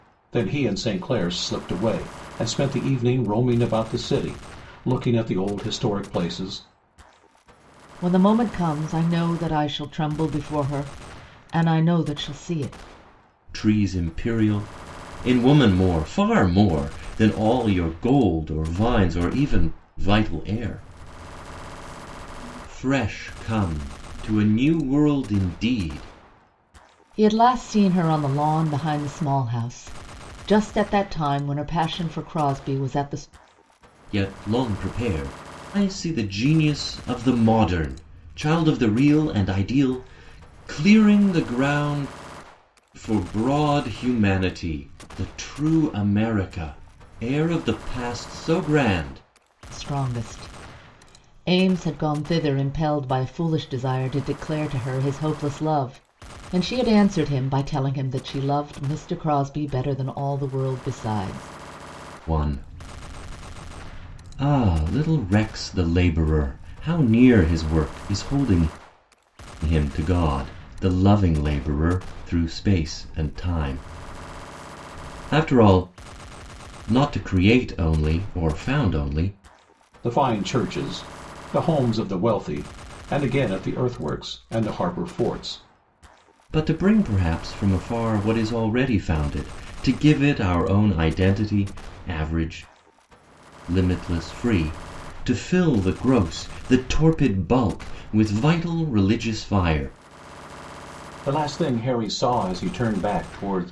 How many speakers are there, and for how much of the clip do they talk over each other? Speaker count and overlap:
3, no overlap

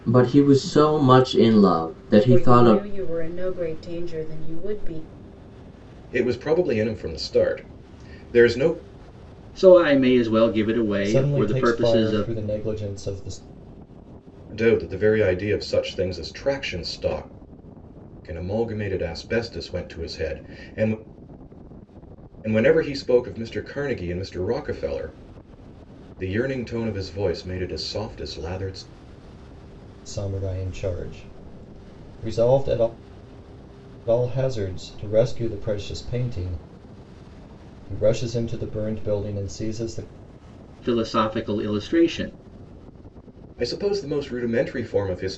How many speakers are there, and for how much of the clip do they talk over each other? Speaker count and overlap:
5, about 4%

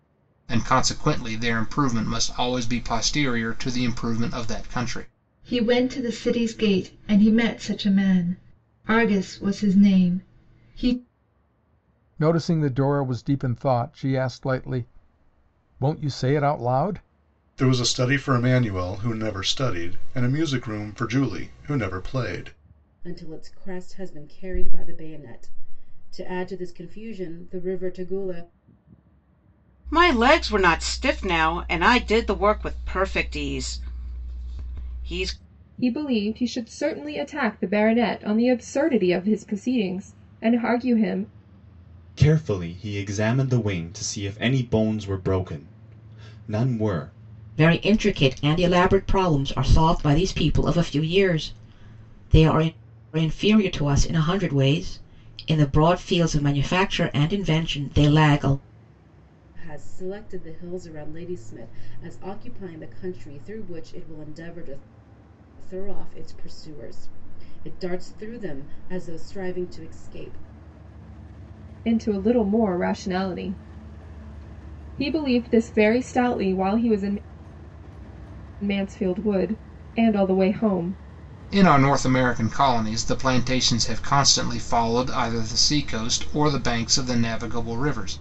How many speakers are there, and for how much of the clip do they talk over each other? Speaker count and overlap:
9, no overlap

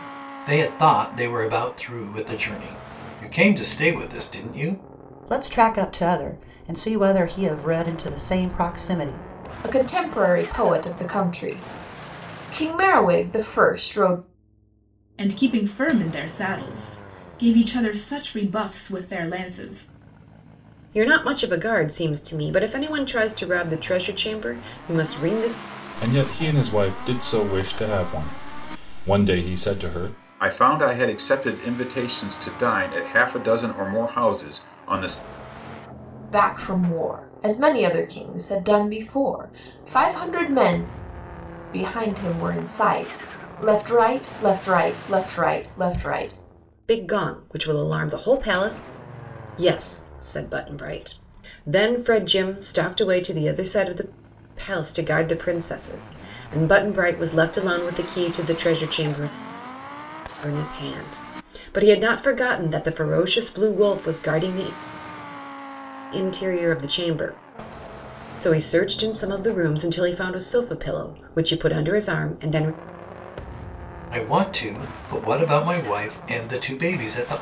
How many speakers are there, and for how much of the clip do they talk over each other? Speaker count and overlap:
7, no overlap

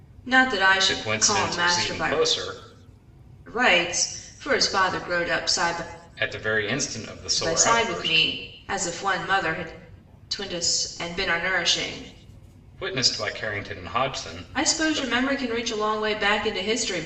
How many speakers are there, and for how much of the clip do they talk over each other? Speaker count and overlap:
2, about 17%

